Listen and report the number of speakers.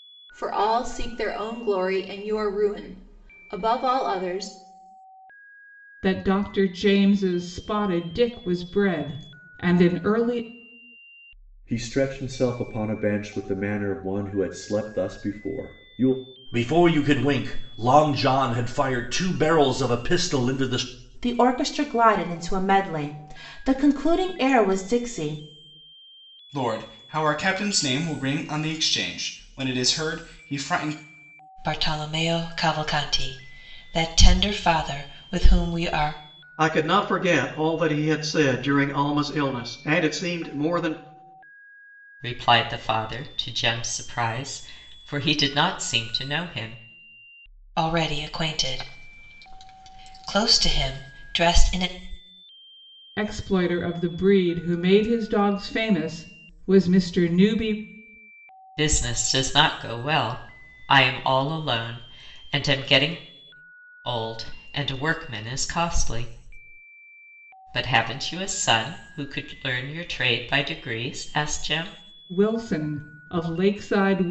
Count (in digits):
9